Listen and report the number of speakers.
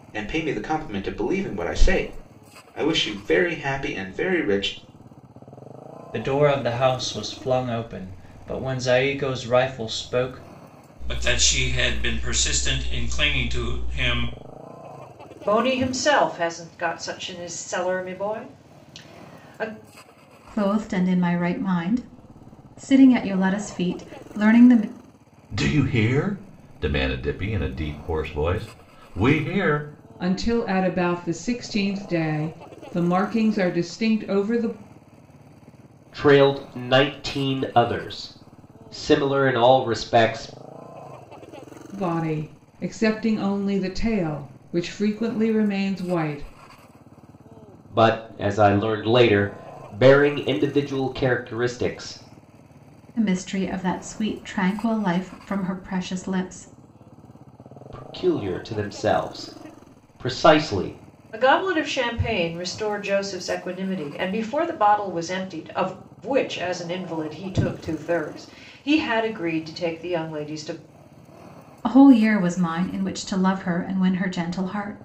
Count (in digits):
8